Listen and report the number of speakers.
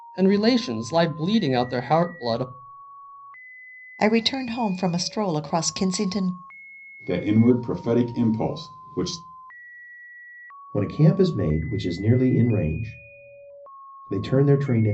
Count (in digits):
4